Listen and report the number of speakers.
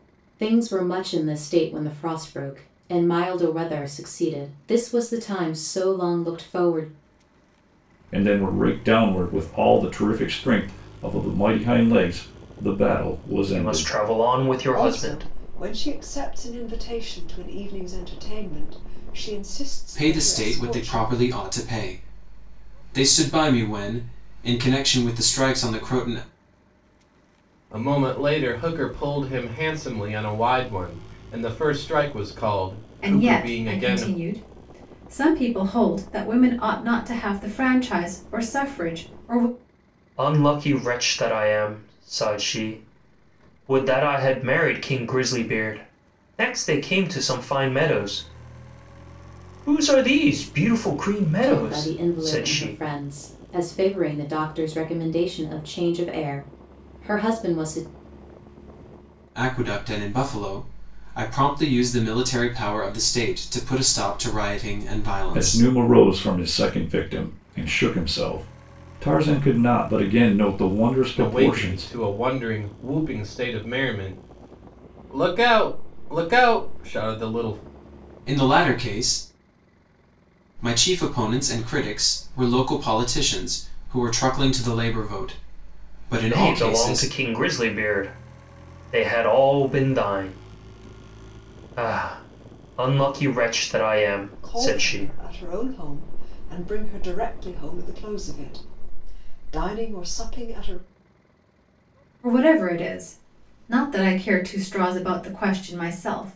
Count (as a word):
seven